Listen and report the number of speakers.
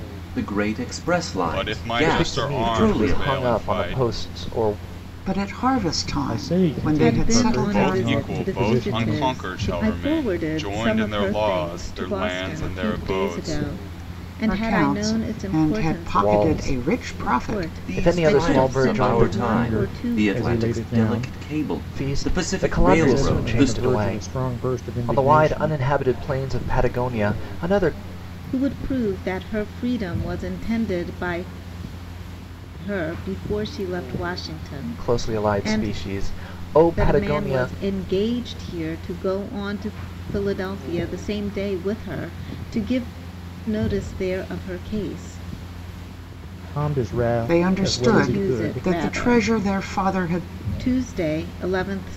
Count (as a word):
six